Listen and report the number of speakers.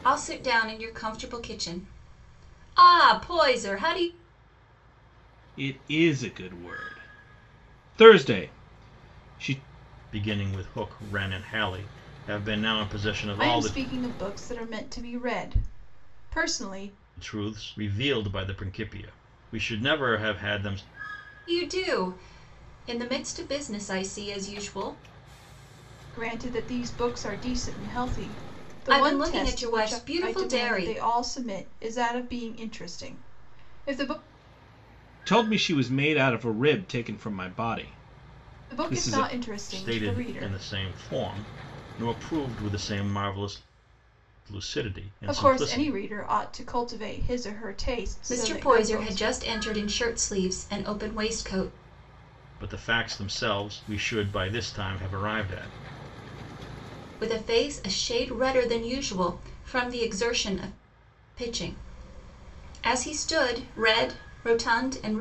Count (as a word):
four